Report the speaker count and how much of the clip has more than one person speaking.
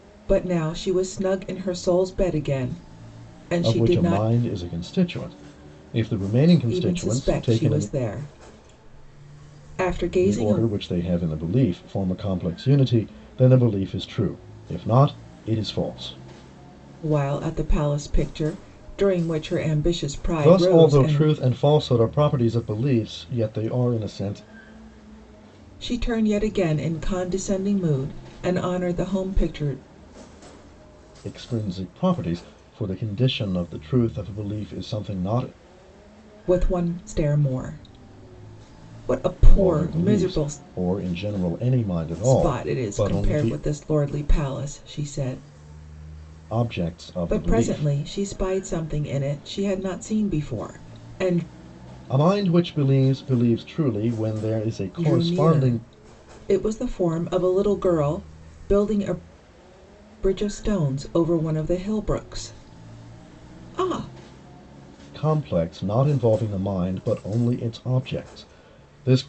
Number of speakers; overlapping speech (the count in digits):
2, about 11%